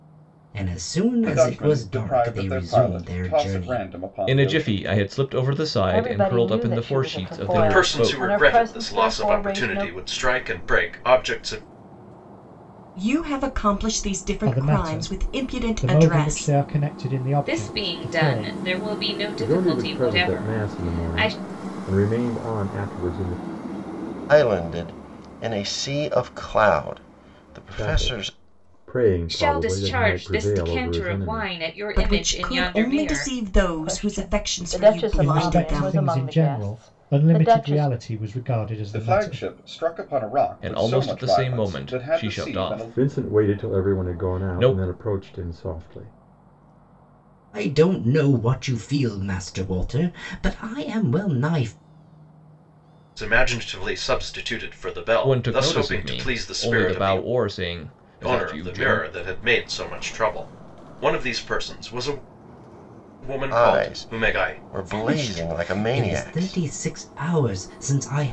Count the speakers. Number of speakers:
10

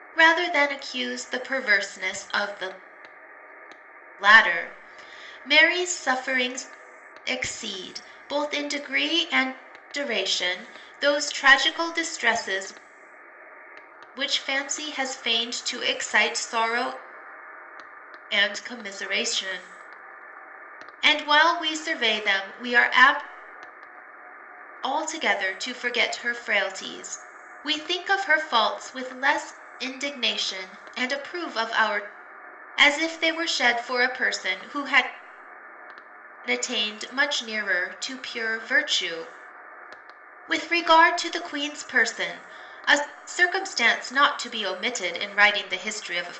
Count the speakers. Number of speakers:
1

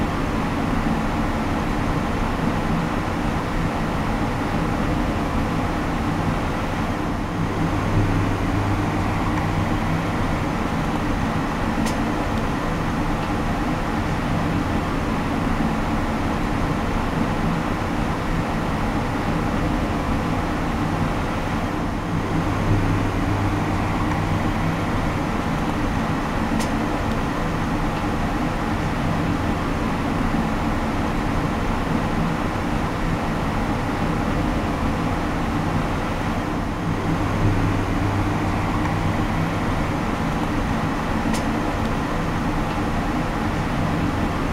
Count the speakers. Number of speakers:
0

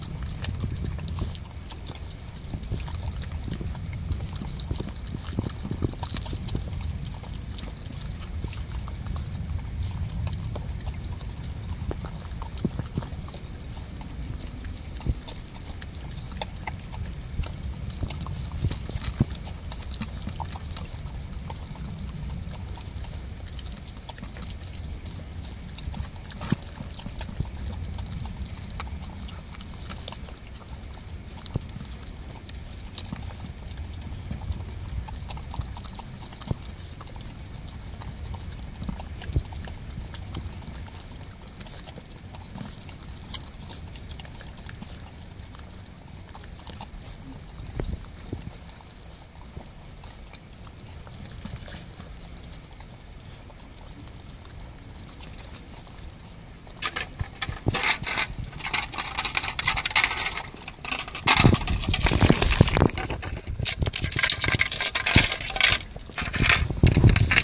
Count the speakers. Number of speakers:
0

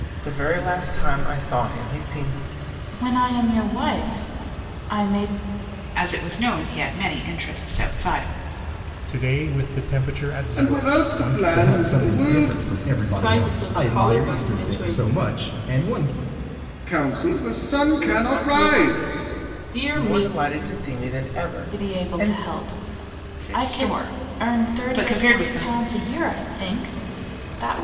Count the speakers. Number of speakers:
7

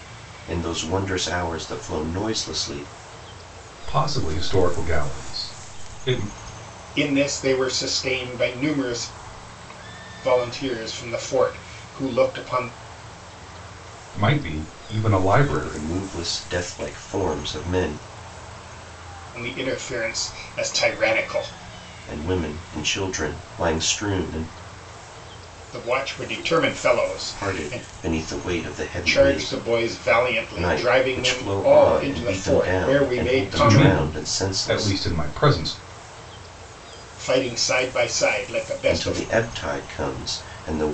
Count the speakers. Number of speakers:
3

